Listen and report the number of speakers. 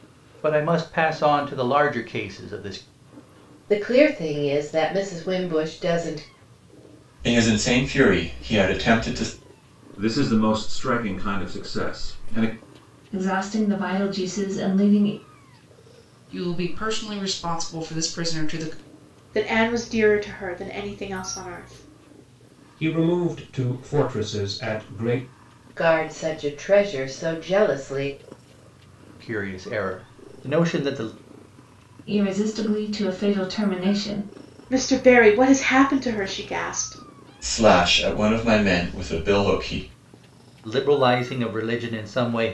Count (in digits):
8